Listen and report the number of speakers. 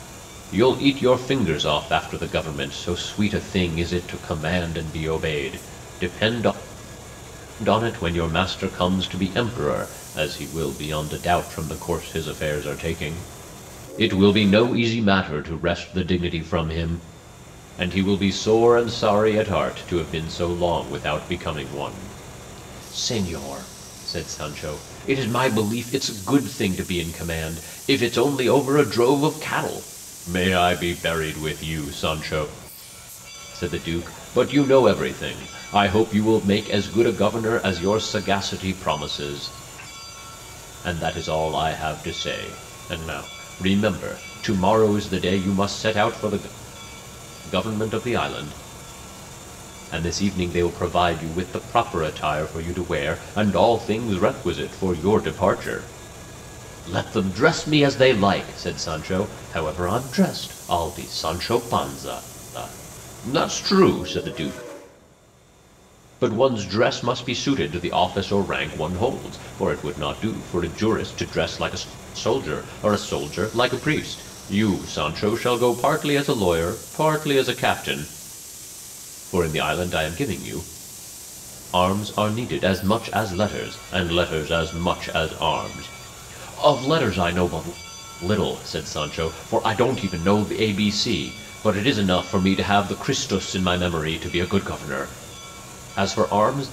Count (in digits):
1